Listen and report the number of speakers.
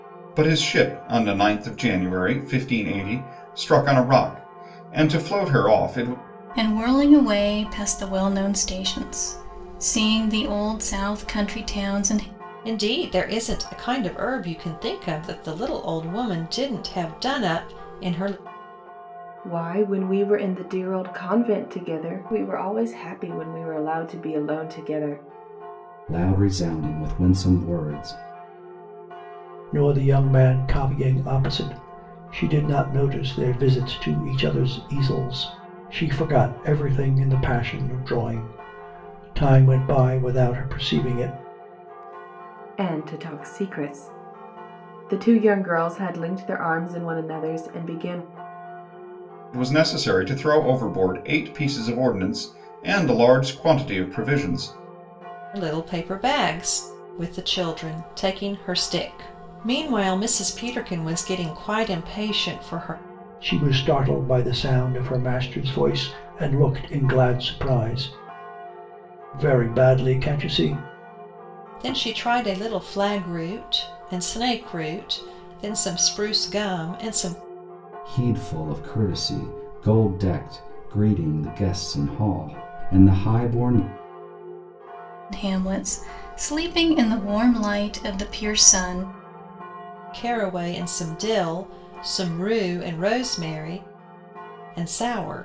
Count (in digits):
6